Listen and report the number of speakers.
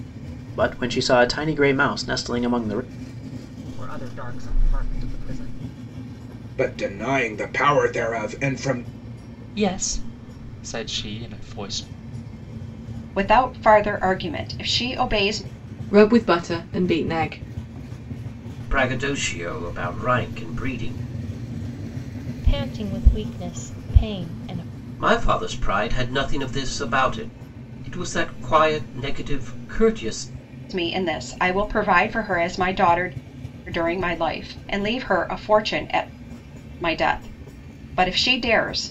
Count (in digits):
8